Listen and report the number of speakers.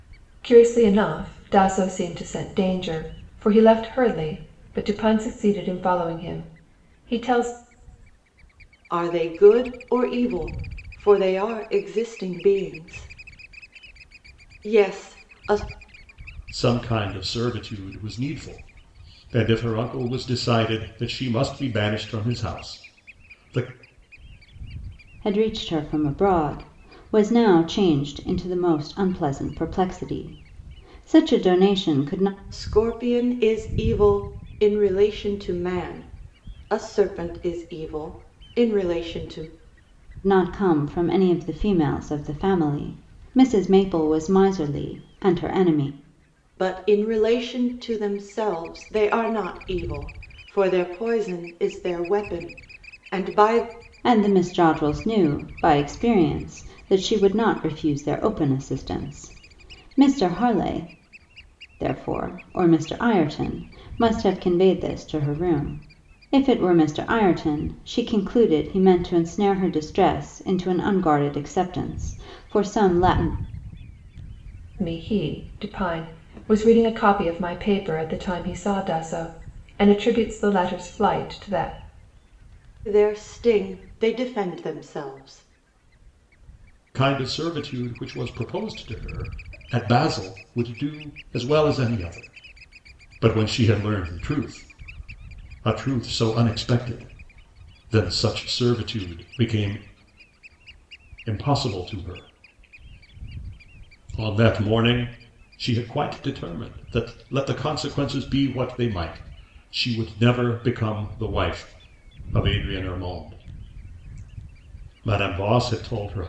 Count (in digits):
4